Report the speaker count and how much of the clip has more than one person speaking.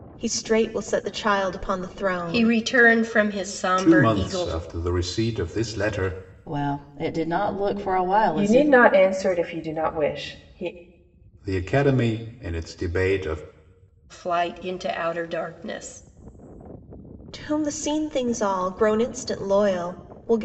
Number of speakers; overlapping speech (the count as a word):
five, about 8%